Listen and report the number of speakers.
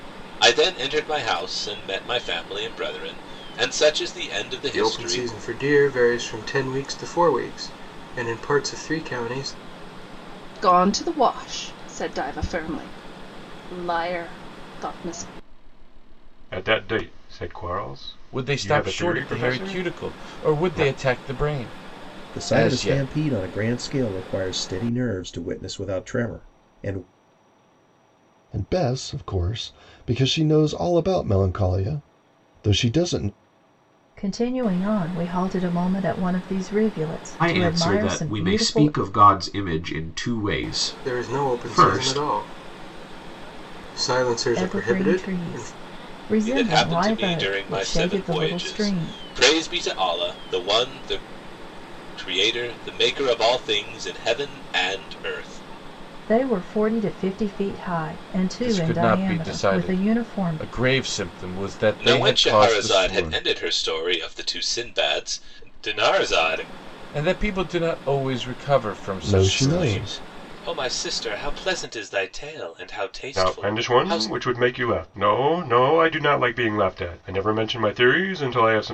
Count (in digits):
9